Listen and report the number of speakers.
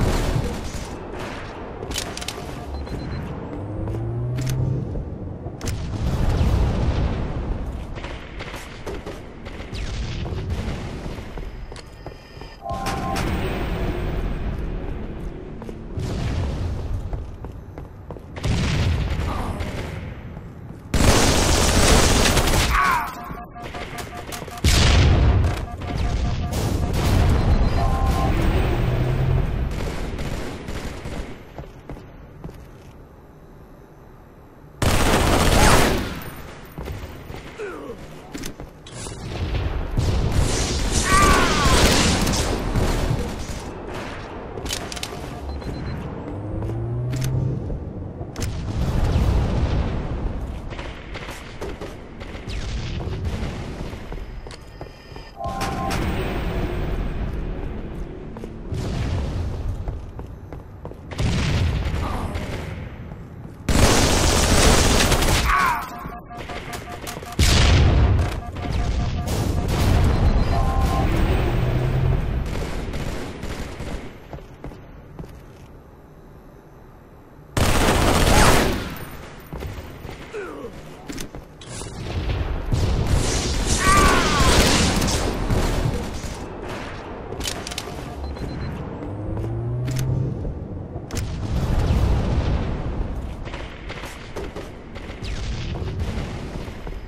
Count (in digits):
0